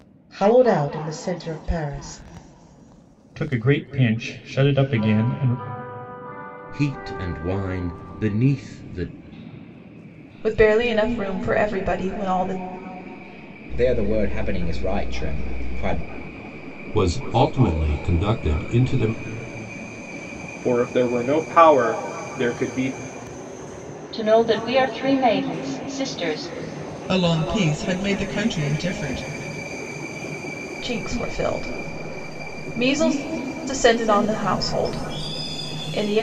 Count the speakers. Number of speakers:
9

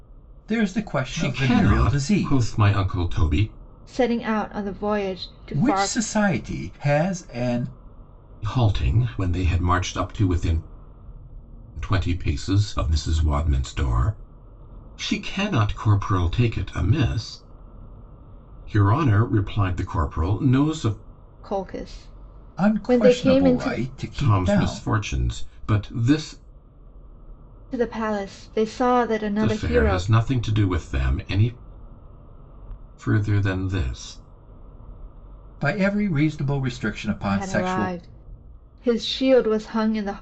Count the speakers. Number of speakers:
3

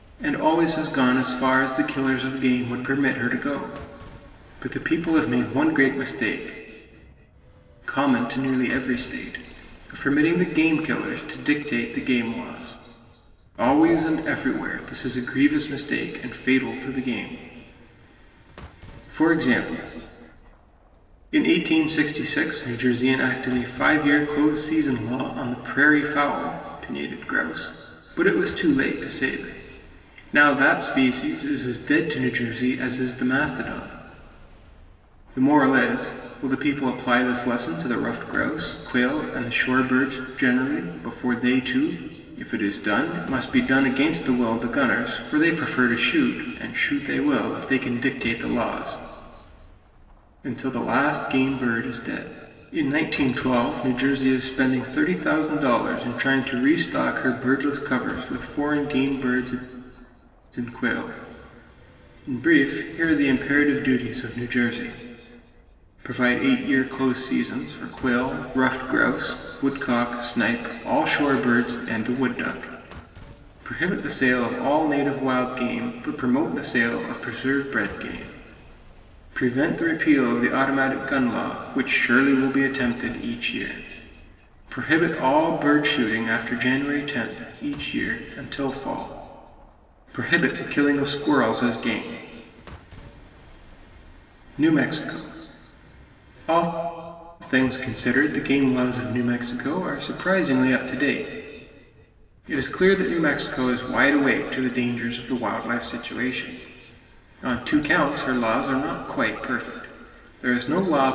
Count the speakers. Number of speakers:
1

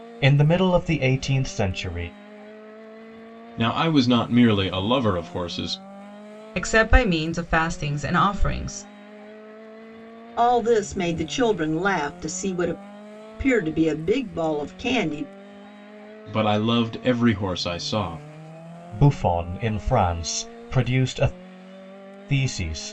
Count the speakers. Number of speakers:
4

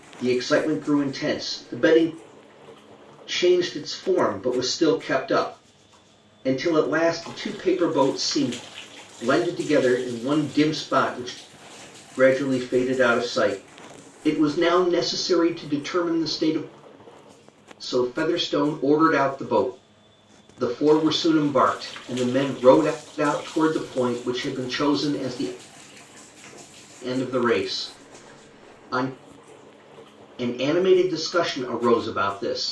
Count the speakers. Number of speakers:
1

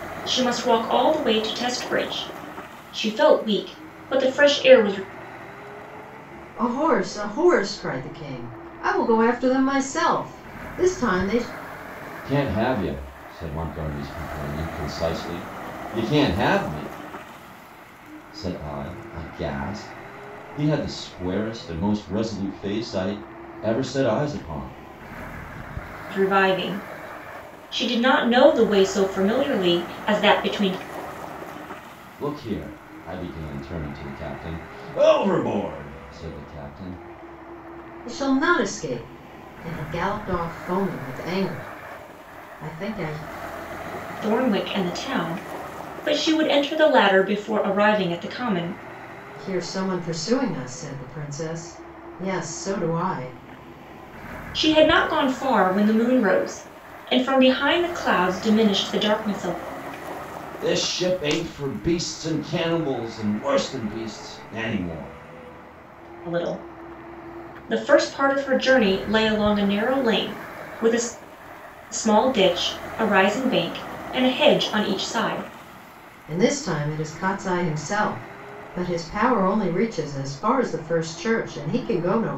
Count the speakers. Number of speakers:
3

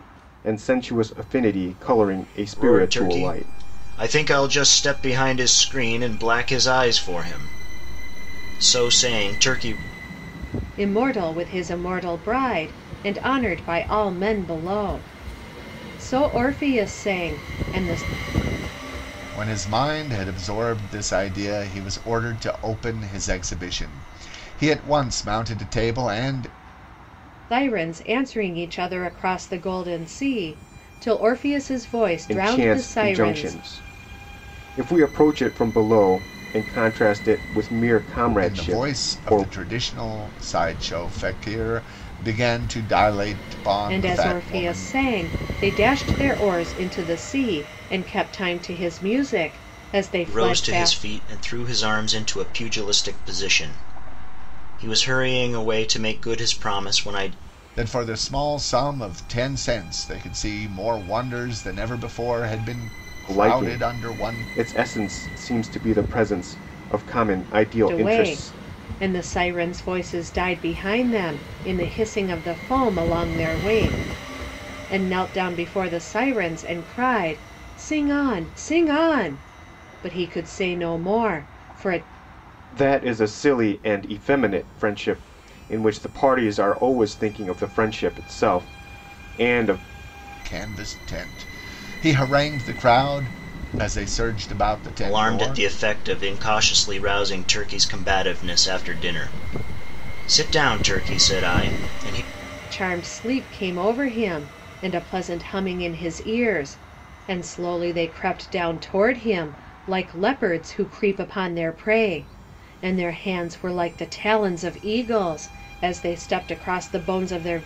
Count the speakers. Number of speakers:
4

